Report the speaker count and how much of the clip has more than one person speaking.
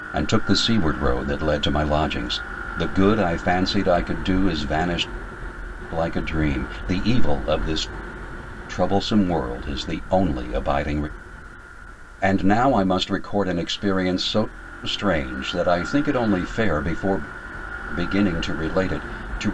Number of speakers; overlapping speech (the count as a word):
one, no overlap